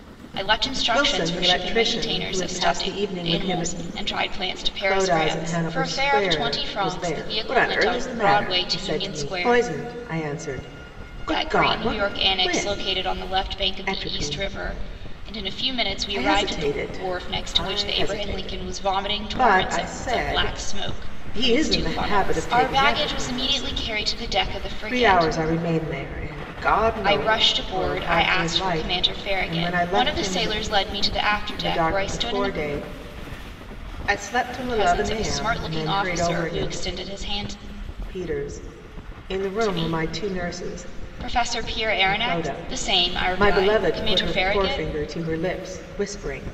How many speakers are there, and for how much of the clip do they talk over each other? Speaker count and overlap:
2, about 61%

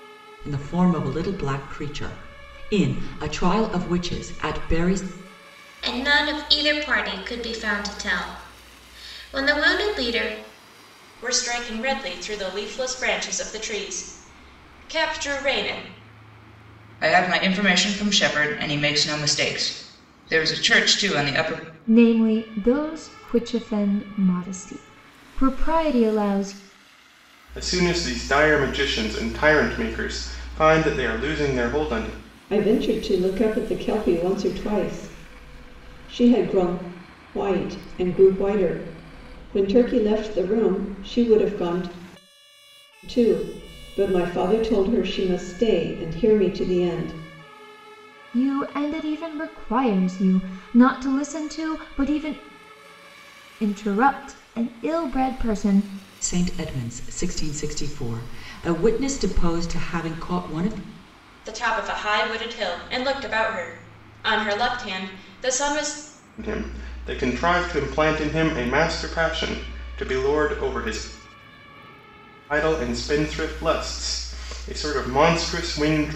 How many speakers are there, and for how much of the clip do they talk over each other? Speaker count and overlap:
7, no overlap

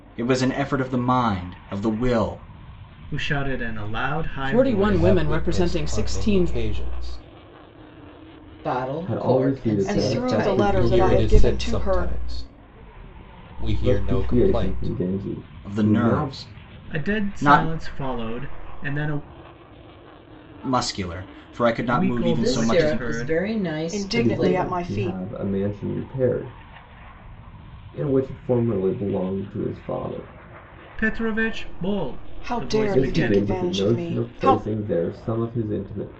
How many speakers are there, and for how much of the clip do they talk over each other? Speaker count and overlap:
7, about 36%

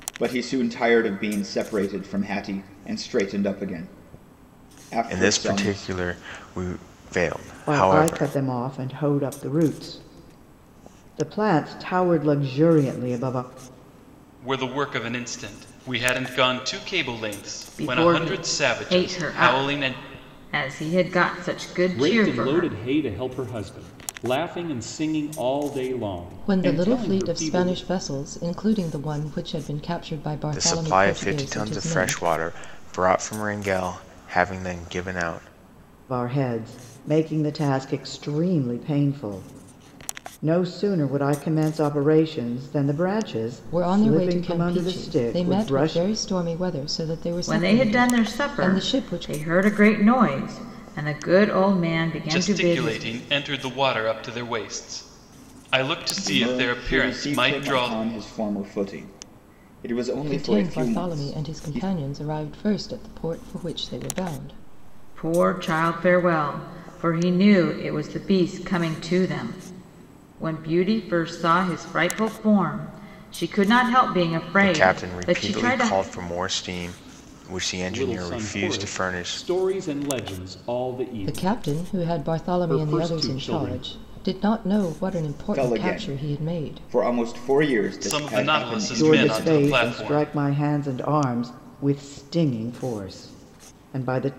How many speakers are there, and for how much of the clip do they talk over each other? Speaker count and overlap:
7, about 27%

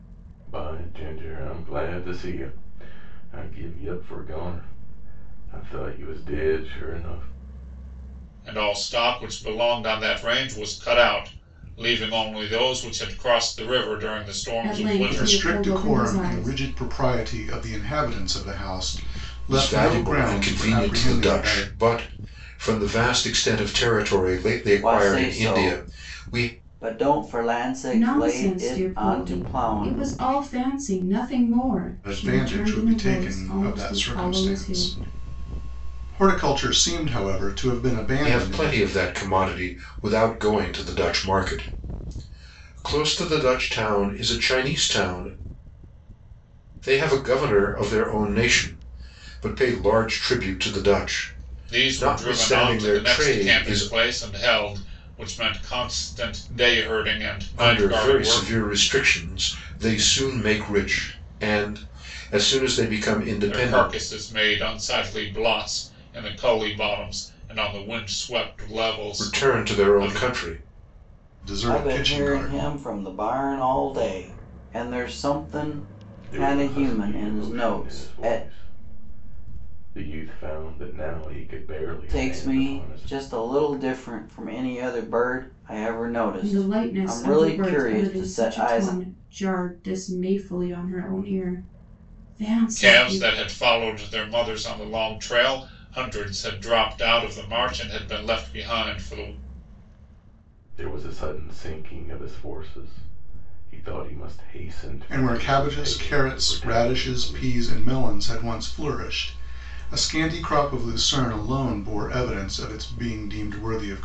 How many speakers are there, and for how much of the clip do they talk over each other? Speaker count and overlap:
6, about 23%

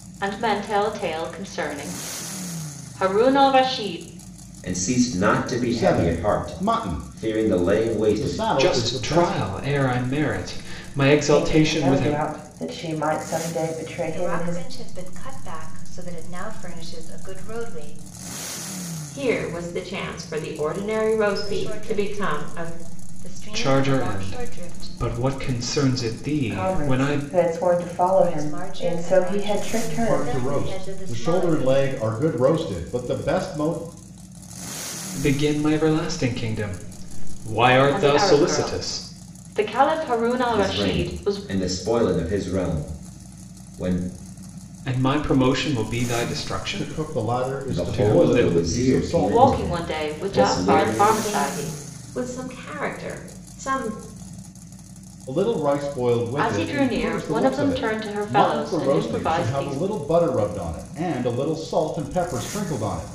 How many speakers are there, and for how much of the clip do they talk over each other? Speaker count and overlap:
7, about 36%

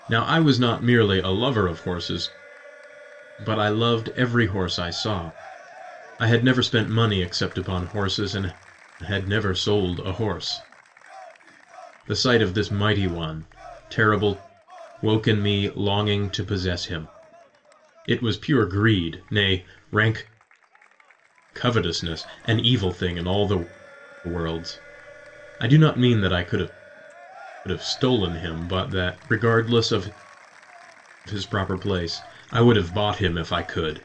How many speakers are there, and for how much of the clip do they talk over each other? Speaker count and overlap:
1, no overlap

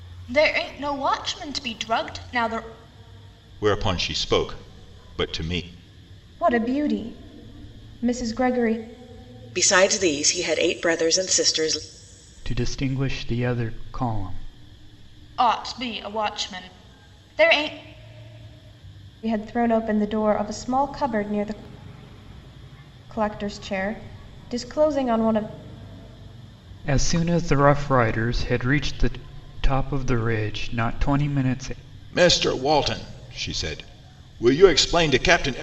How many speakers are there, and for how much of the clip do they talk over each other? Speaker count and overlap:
5, no overlap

